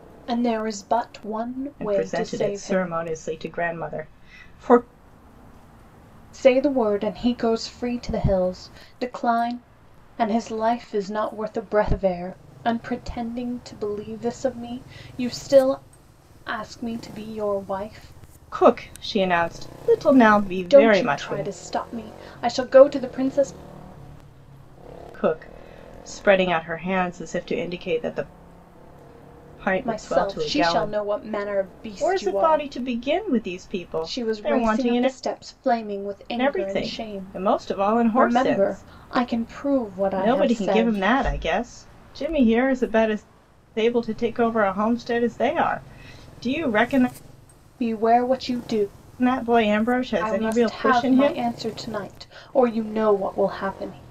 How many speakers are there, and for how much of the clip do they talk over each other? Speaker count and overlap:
two, about 17%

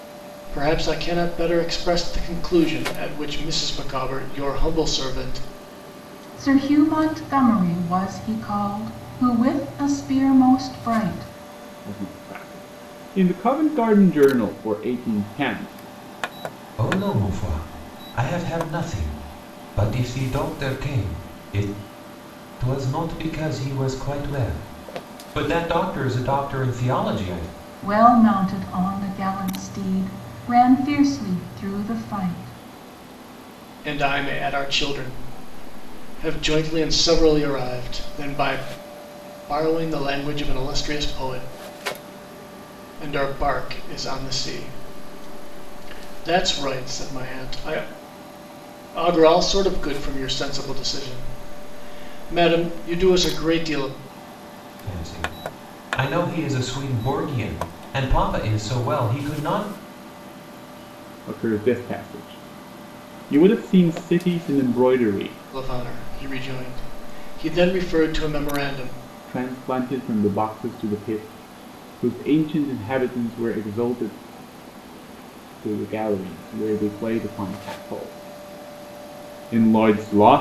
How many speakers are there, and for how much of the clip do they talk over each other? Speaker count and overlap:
four, no overlap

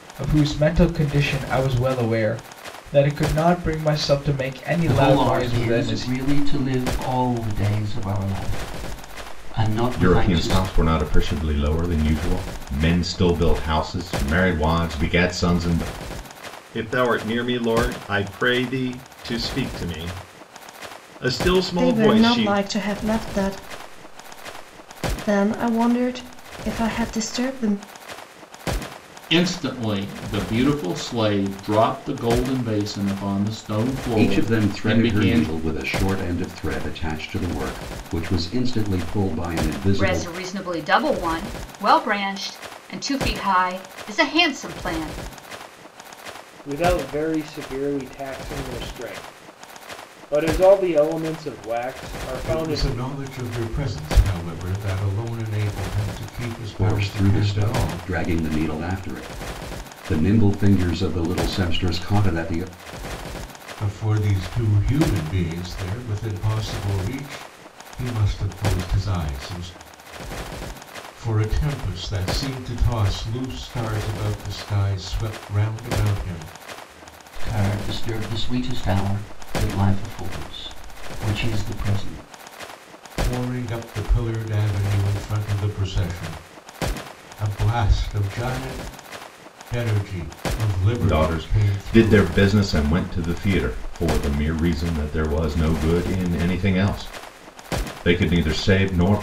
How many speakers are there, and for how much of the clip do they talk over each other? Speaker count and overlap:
ten, about 8%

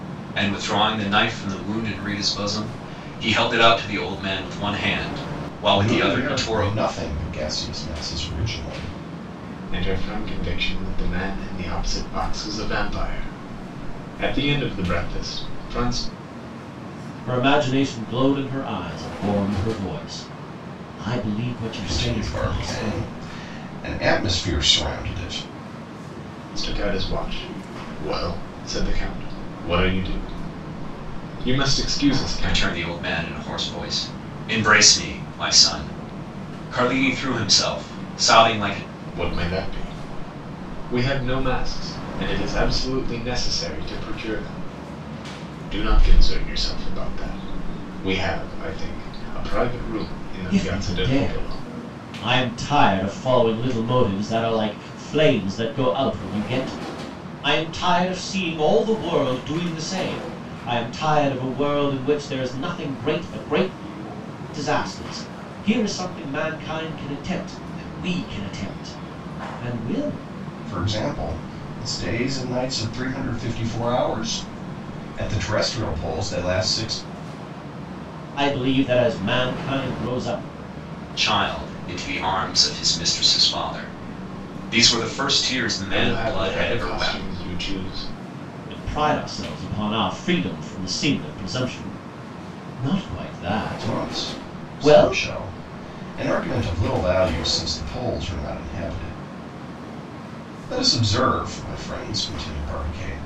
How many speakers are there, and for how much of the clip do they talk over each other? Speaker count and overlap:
four, about 6%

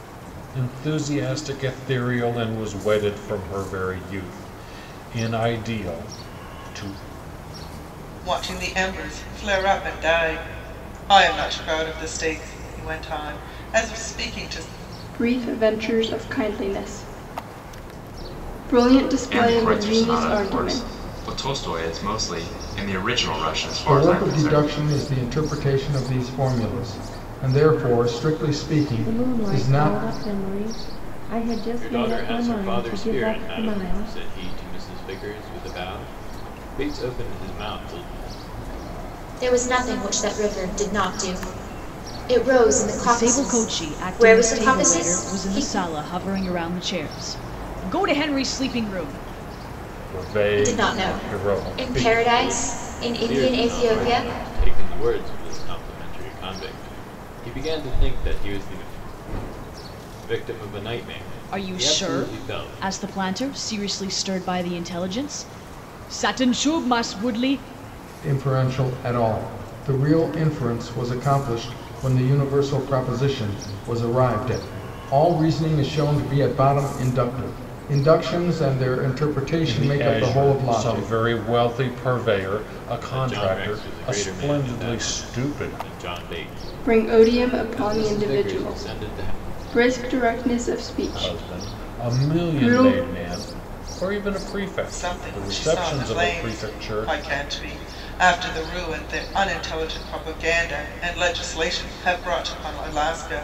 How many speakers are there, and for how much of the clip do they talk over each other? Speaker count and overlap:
nine, about 24%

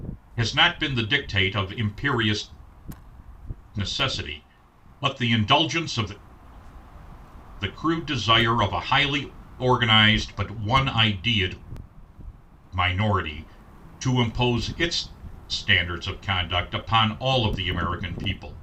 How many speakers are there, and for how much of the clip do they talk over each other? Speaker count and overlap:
one, no overlap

